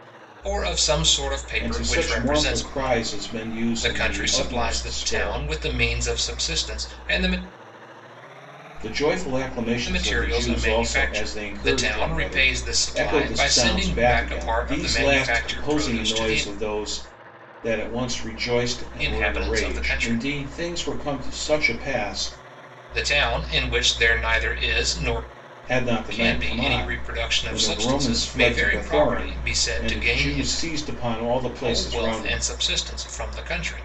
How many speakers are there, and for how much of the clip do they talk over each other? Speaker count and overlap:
two, about 50%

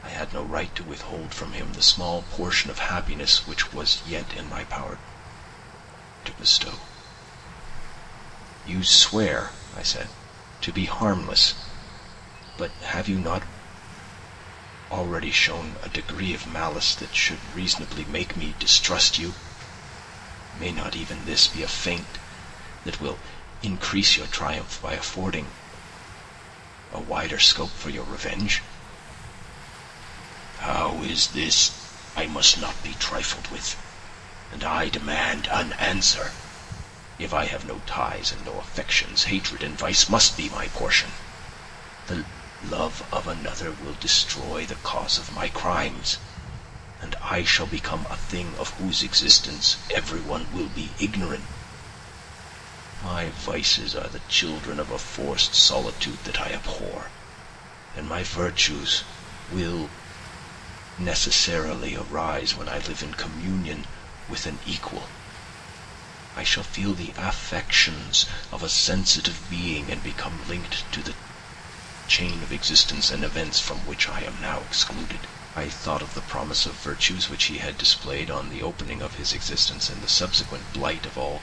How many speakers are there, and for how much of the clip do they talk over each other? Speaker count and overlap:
one, no overlap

